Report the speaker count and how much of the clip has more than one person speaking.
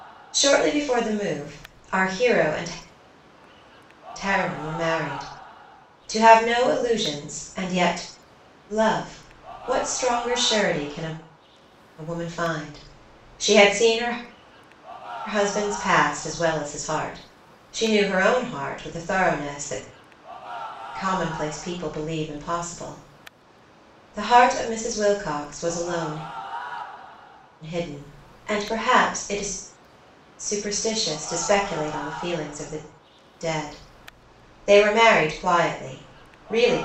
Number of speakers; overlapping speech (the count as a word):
one, no overlap